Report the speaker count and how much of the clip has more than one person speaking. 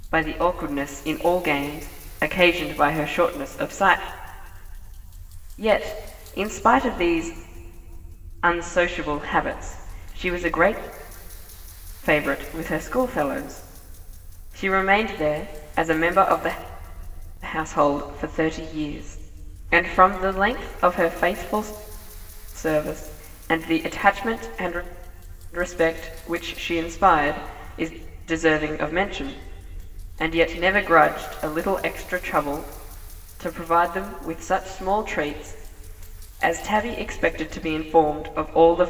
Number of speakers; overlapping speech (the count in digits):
1, no overlap